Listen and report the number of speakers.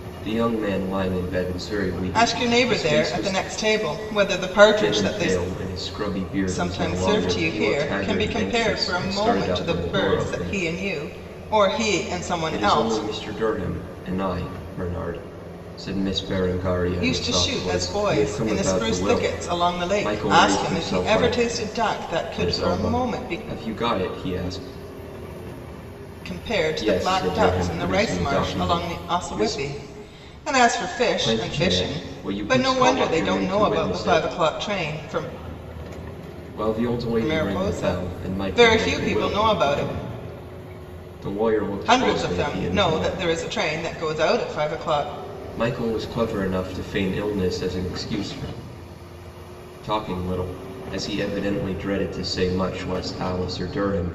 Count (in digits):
2